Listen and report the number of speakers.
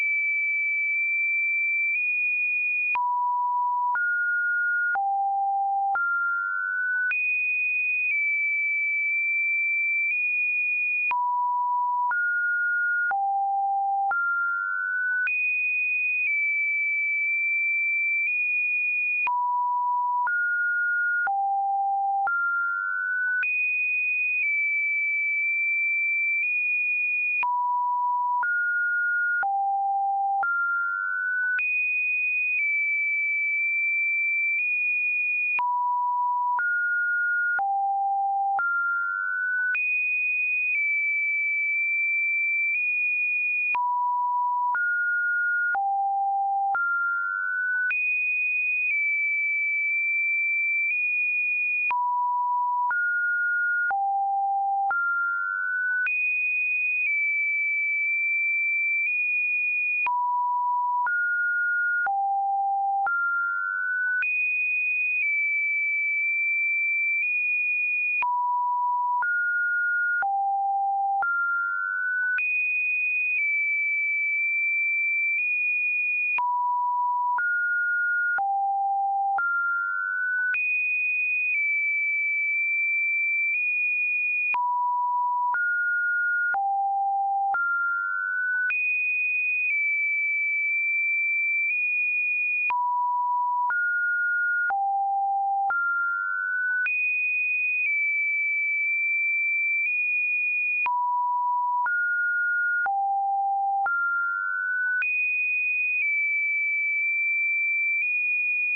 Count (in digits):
0